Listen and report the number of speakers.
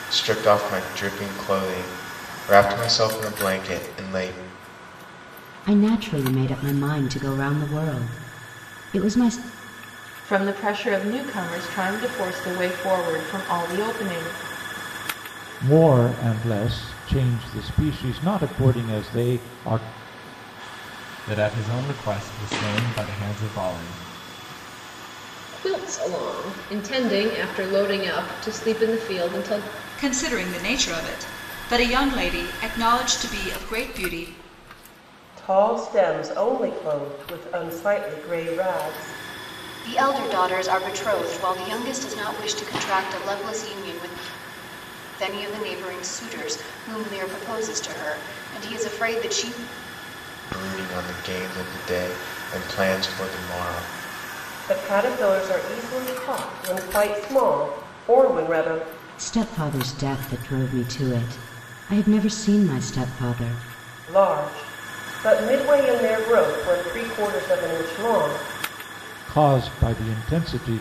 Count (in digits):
9